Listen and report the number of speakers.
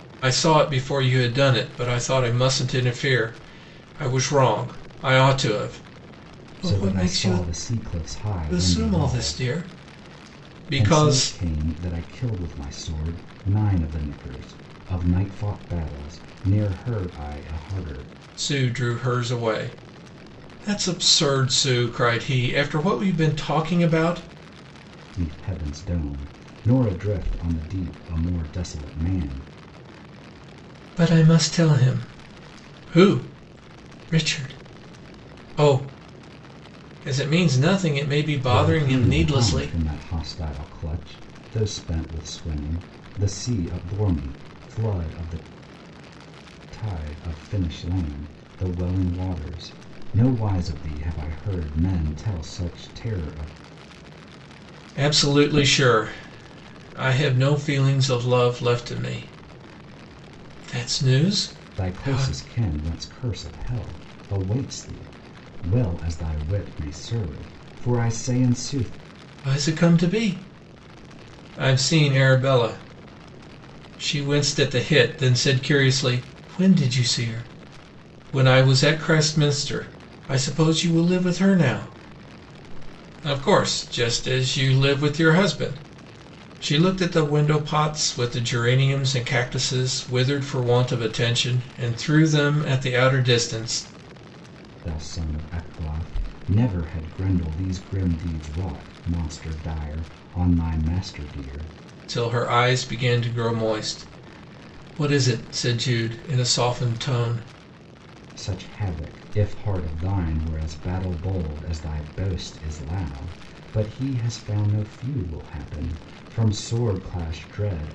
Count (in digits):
2